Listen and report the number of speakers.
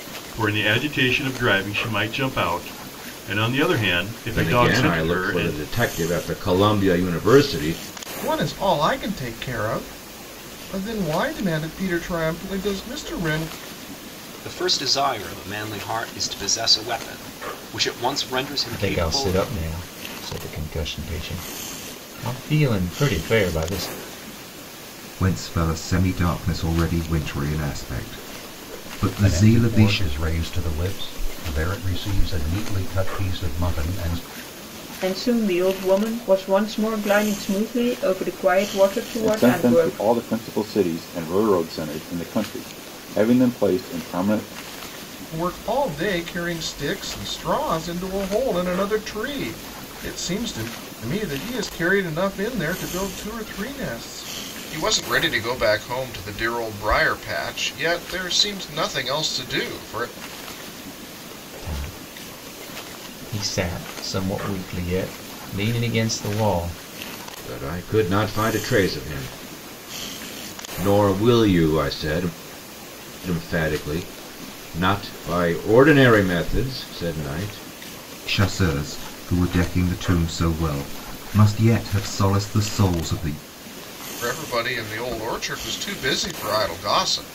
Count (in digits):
9